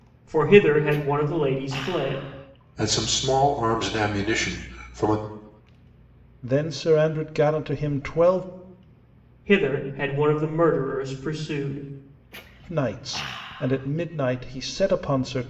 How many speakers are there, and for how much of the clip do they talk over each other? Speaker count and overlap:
three, no overlap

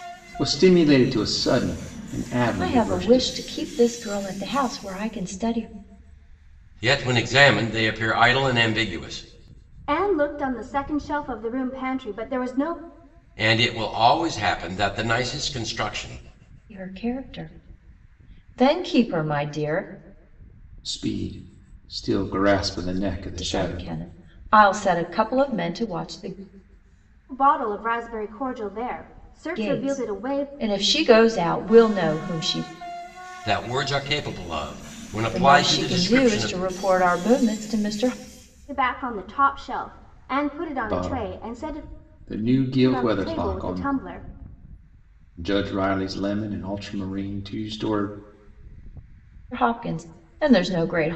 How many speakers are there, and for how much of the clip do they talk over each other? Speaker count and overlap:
four, about 11%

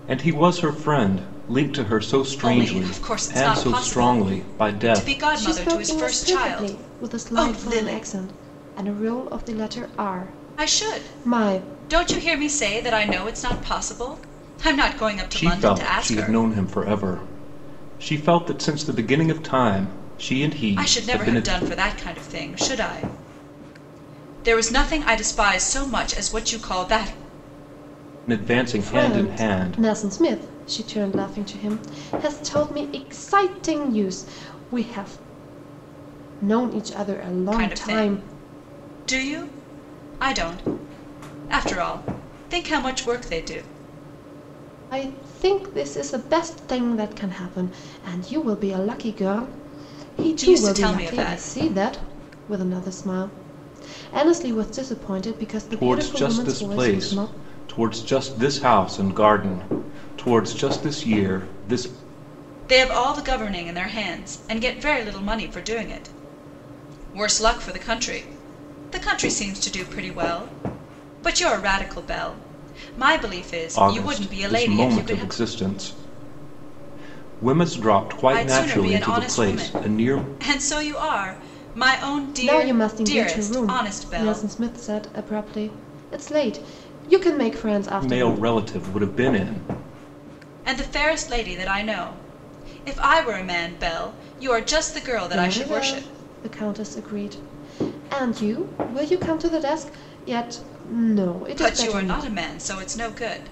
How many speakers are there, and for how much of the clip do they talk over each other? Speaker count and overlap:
three, about 20%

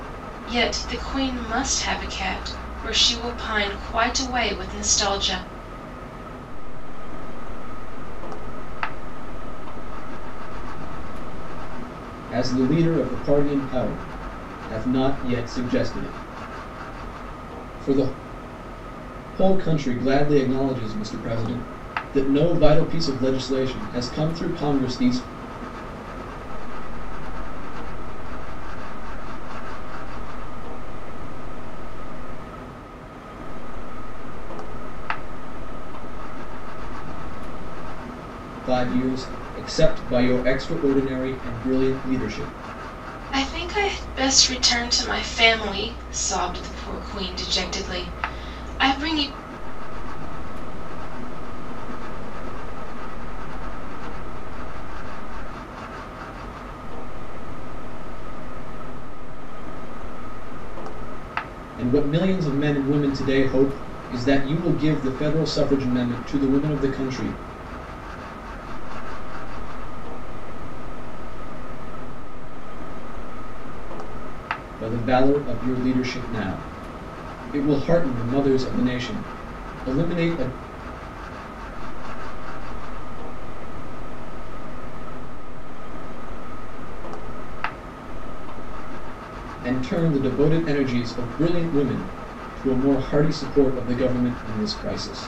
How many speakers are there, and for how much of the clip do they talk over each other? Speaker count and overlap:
three, no overlap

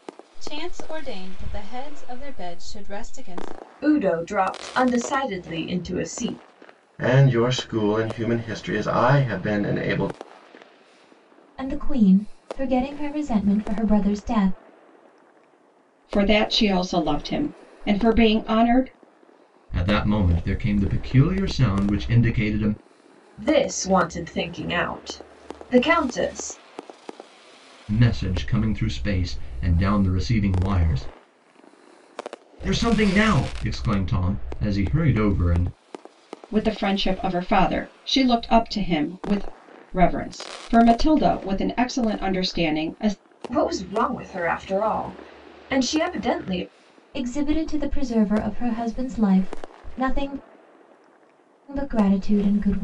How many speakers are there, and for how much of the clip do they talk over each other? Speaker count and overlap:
six, no overlap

